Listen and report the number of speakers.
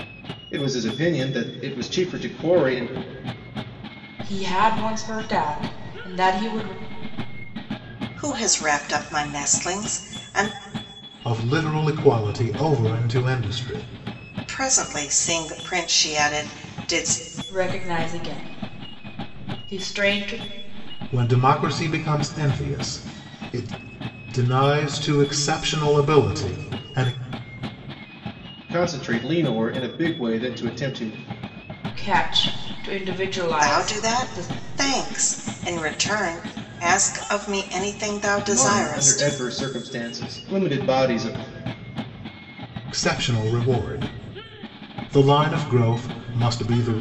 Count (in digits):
4